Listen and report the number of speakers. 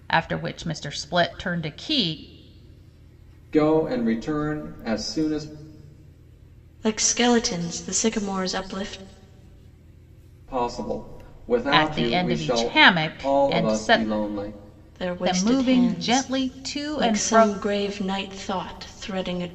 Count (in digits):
3